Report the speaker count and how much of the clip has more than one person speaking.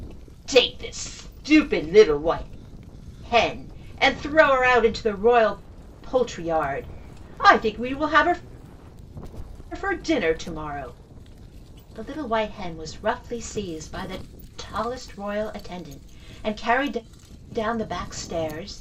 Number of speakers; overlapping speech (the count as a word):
one, no overlap